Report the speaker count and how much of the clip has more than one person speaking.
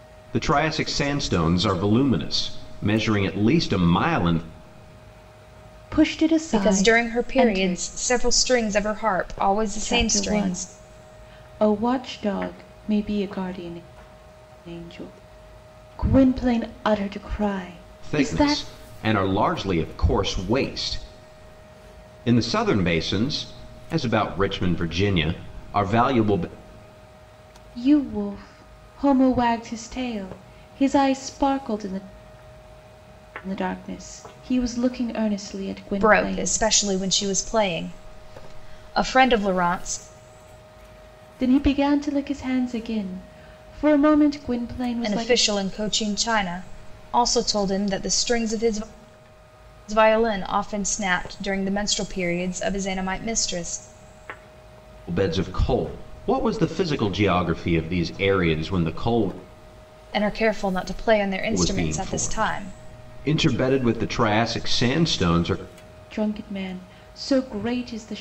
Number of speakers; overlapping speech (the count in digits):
3, about 8%